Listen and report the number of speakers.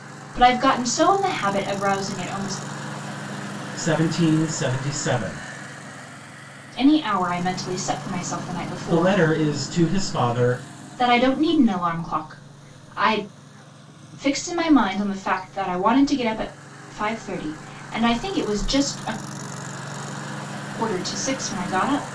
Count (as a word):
two